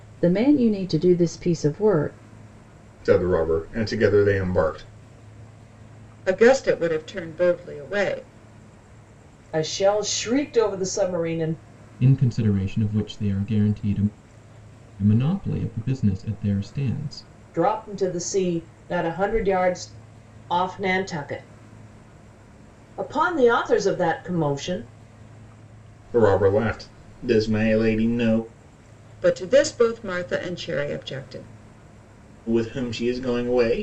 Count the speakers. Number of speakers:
5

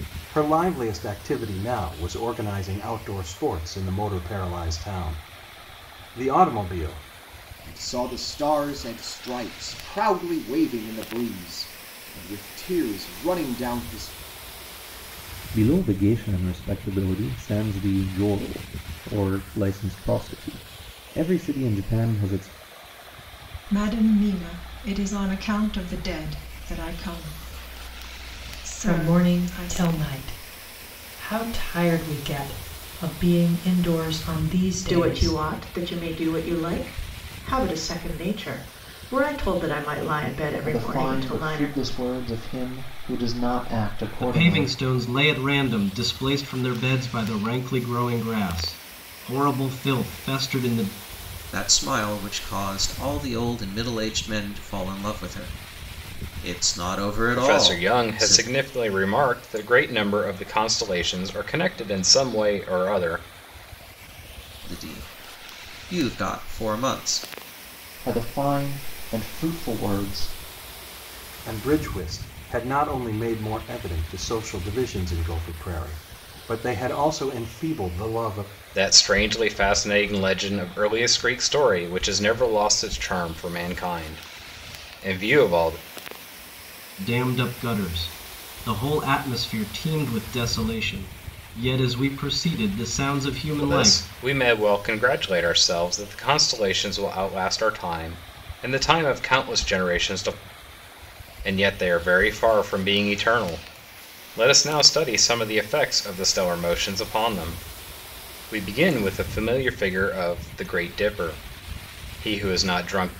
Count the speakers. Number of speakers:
10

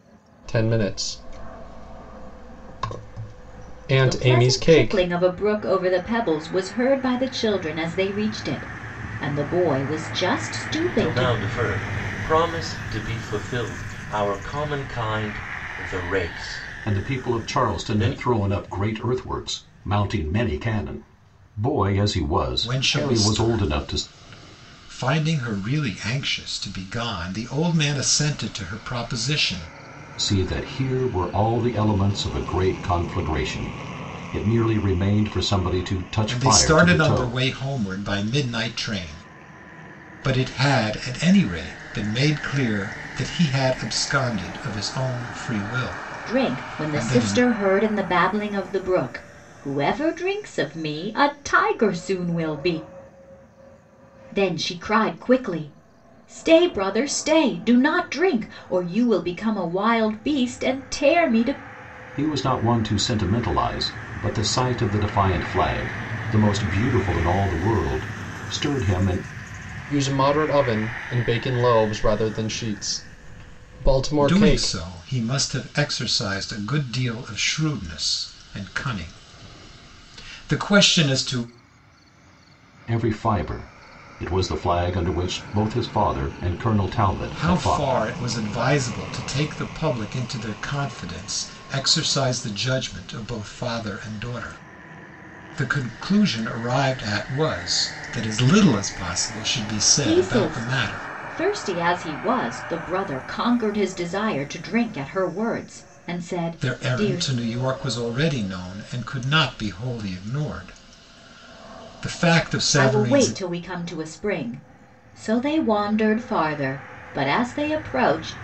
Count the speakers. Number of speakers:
5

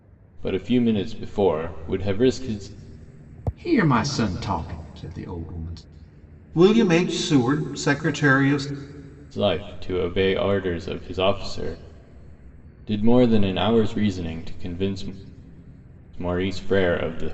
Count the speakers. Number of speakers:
3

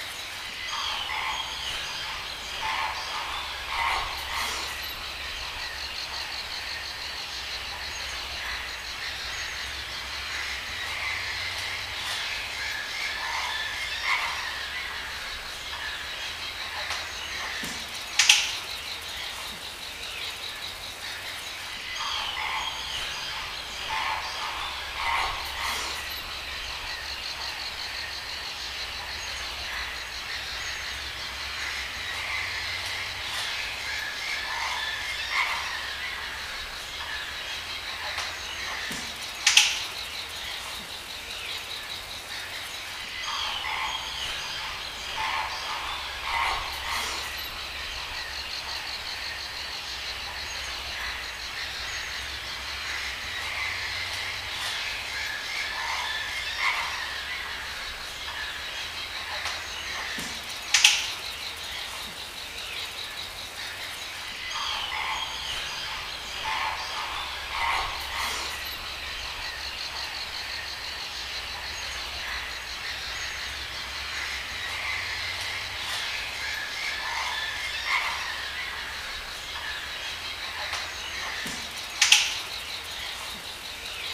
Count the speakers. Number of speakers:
0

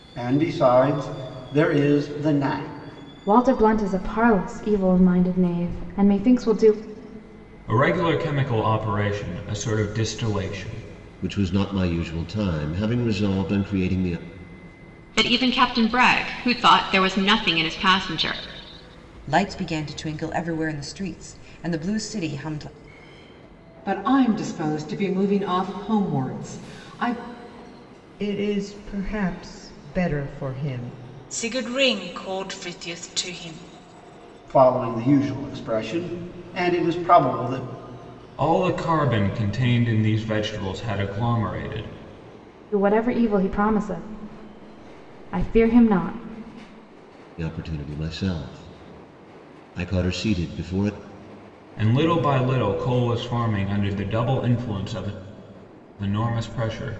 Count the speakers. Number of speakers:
9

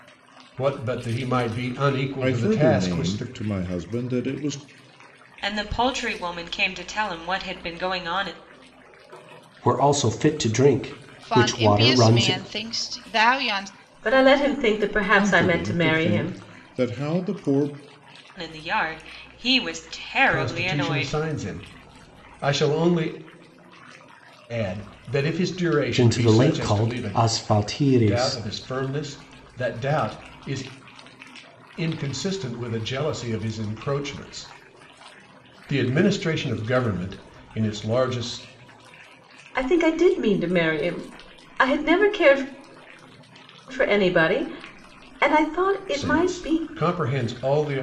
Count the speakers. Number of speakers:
6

